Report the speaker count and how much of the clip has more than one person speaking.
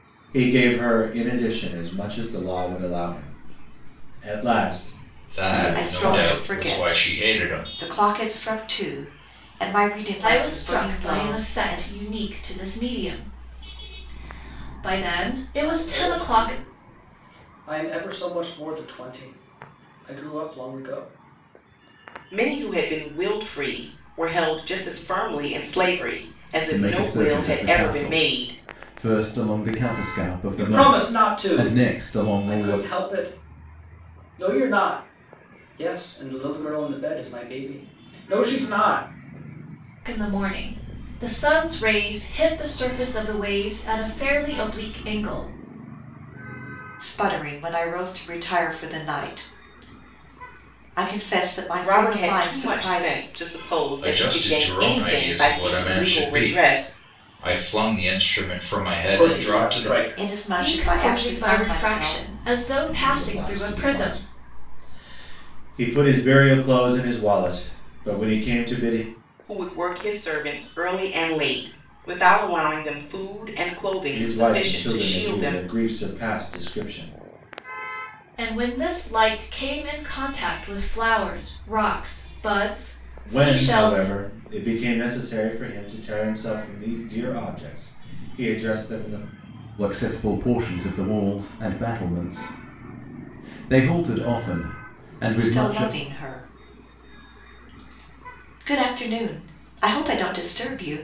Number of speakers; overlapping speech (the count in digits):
7, about 21%